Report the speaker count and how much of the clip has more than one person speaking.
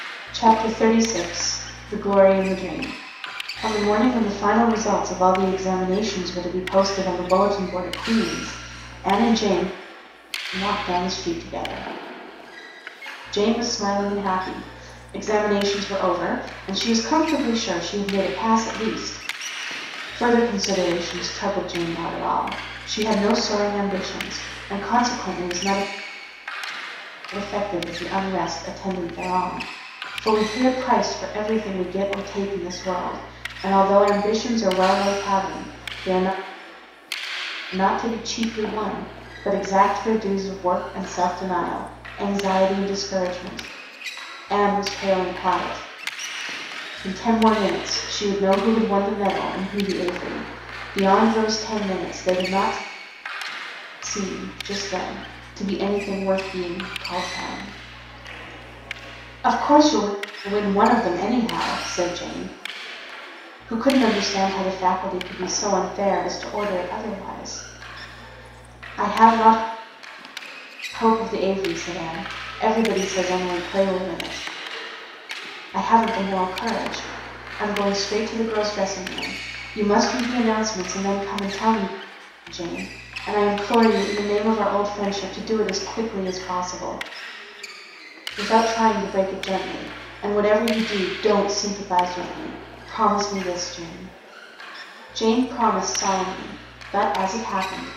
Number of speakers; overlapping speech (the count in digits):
1, no overlap